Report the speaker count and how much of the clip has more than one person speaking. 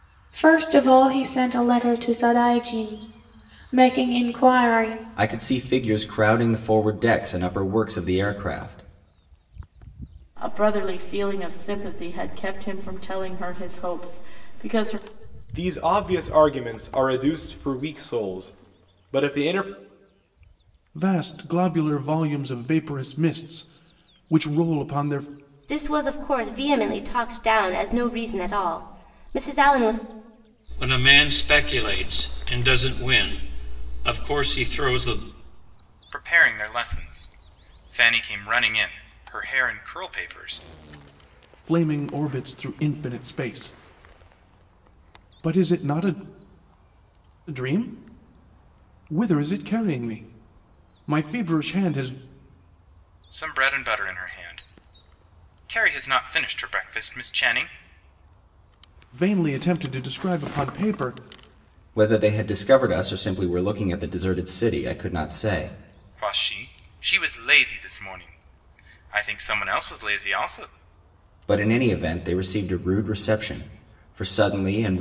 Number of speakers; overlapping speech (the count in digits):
8, no overlap